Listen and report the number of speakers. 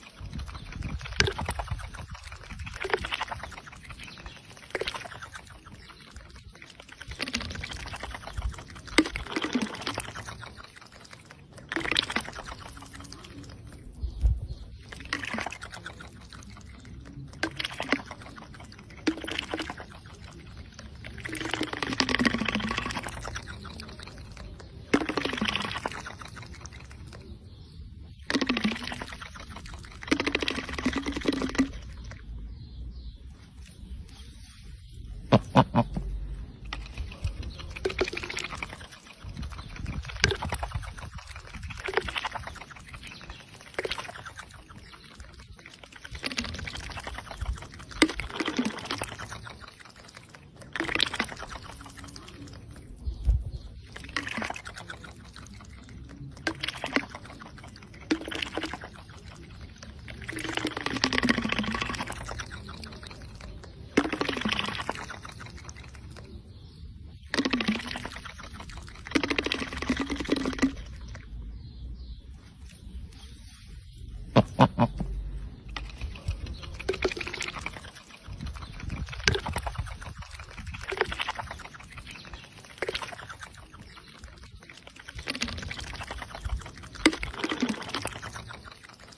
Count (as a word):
zero